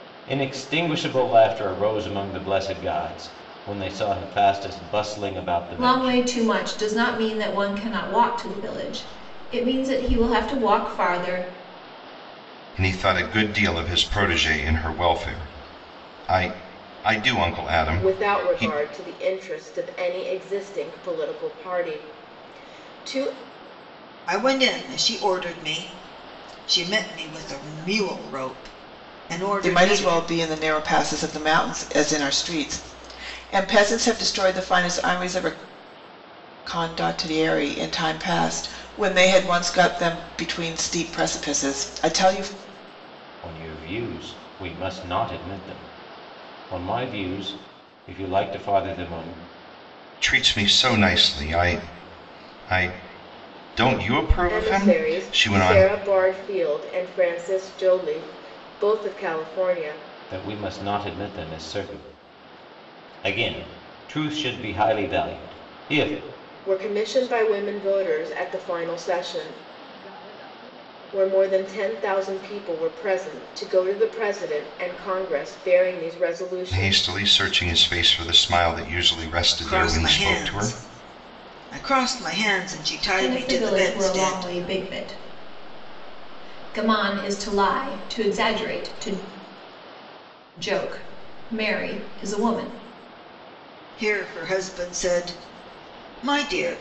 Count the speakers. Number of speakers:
six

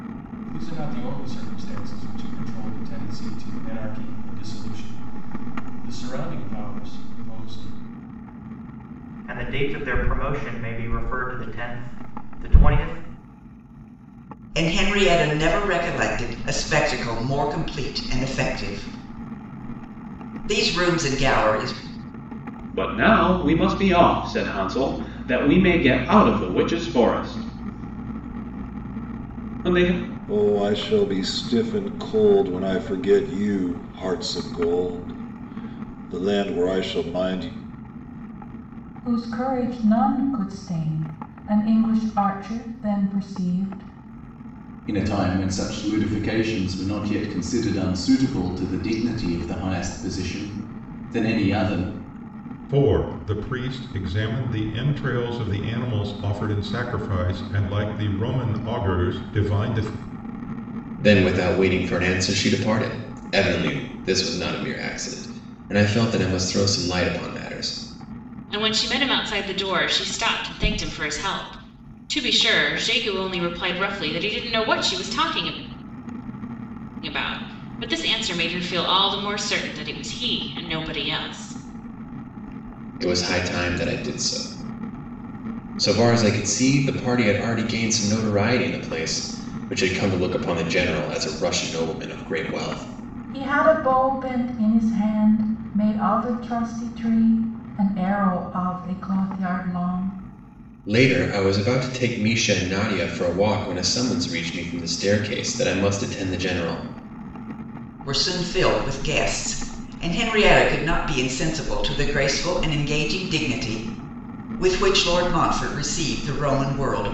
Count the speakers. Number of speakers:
ten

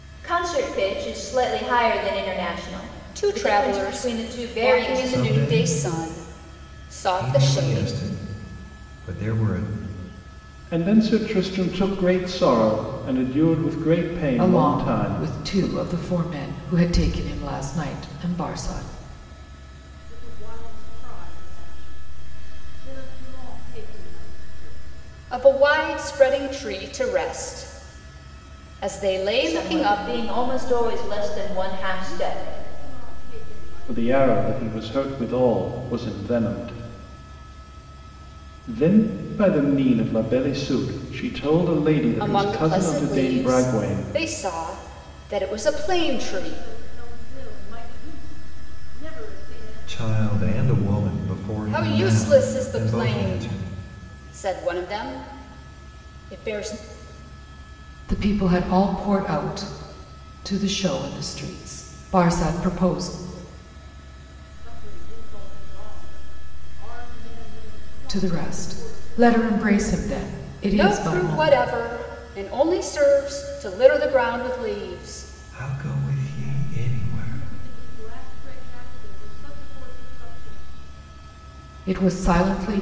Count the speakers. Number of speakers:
six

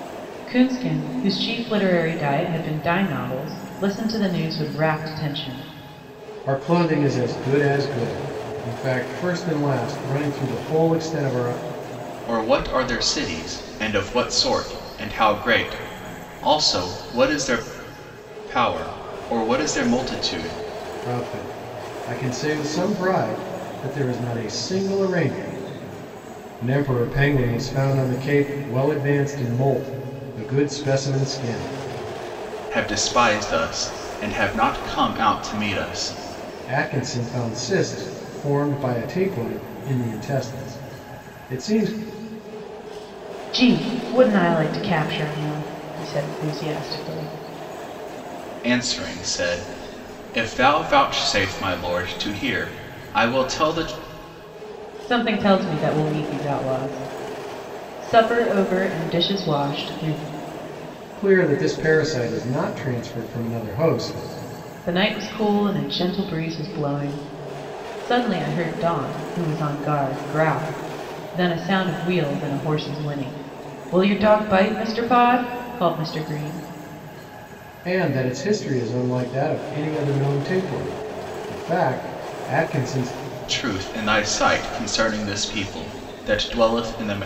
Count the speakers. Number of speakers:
three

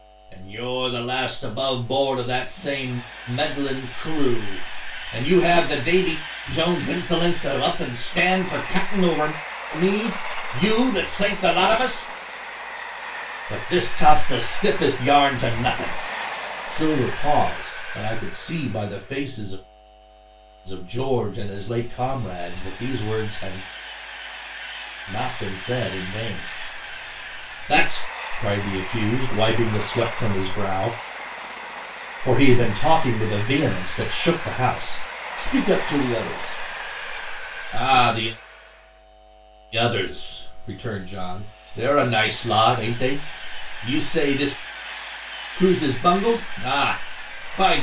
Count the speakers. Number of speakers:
one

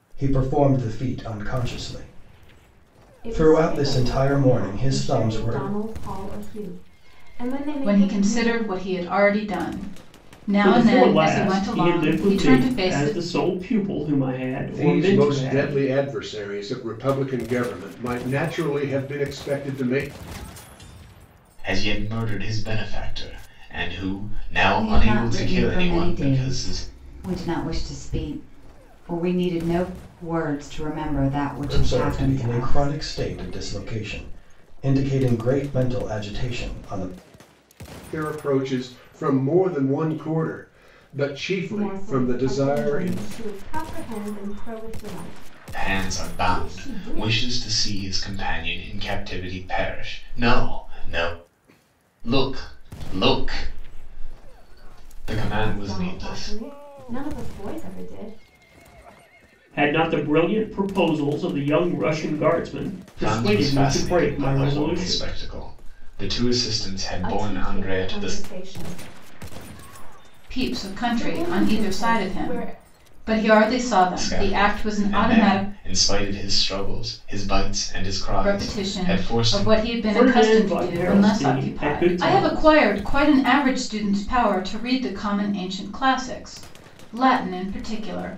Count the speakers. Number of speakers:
seven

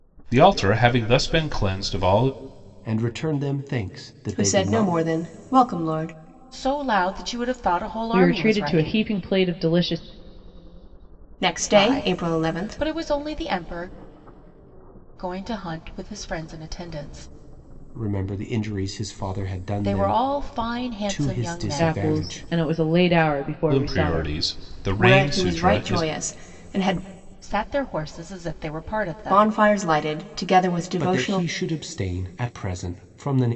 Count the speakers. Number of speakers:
five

